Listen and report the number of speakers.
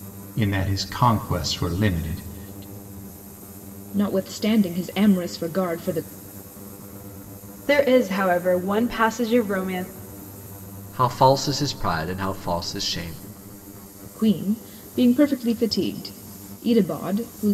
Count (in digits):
4